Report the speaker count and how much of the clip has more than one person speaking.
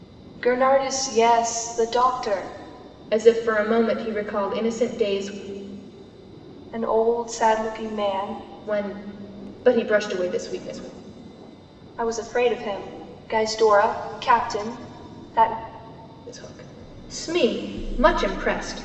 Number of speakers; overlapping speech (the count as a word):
two, no overlap